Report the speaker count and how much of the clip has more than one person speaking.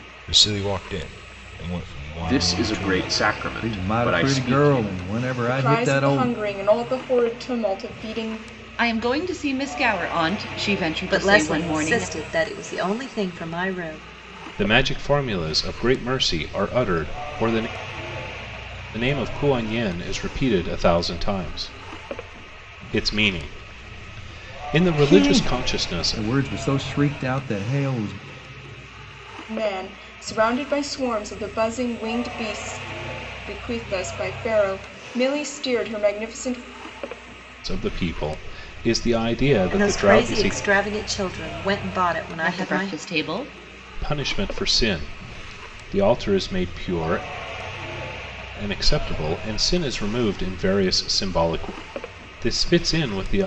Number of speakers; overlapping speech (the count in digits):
7, about 14%